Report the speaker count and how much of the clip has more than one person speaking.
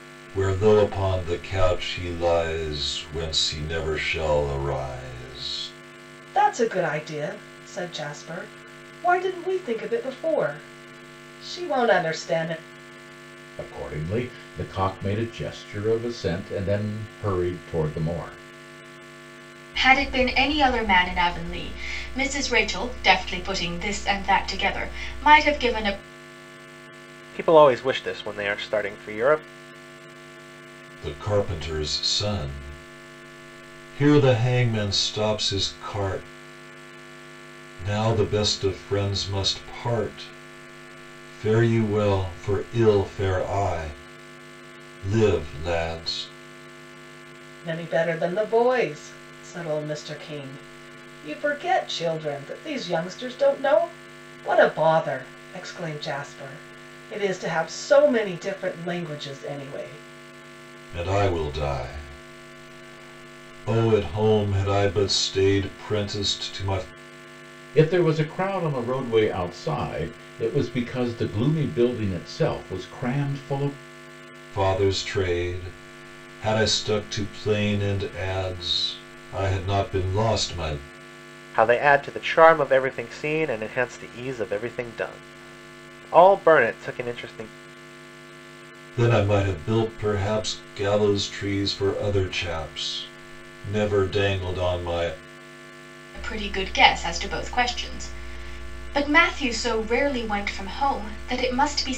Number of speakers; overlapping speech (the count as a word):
five, no overlap